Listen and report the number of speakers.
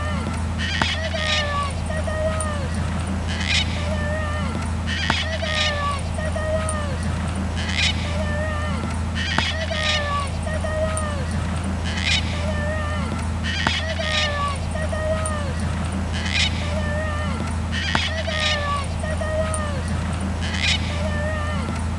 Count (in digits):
0